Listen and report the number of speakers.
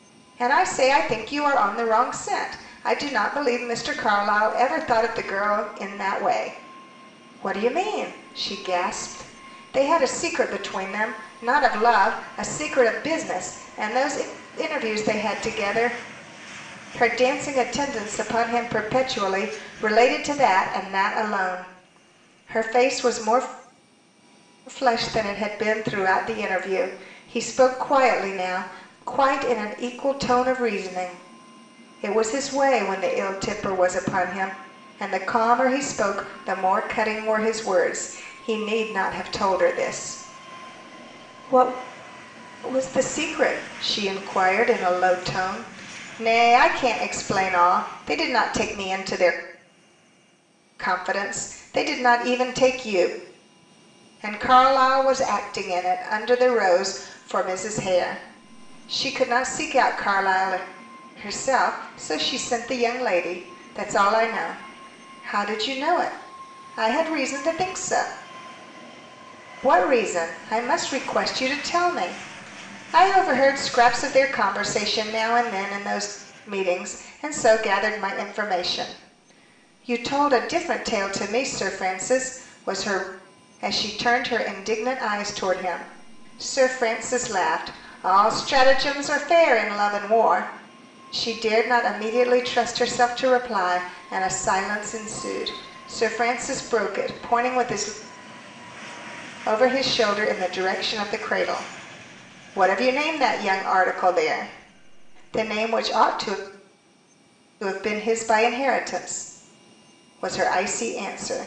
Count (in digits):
1